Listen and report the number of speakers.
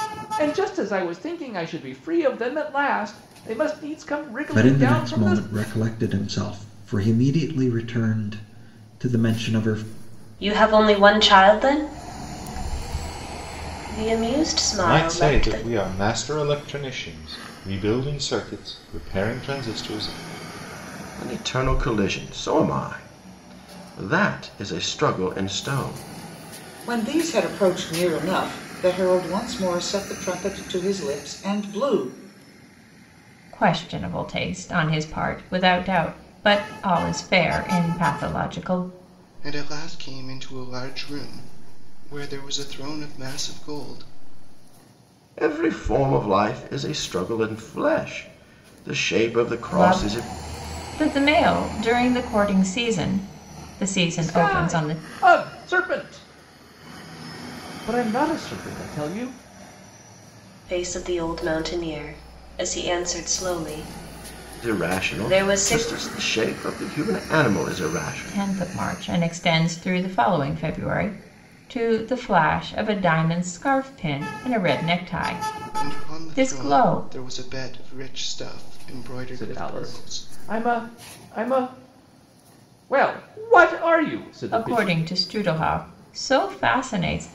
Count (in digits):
8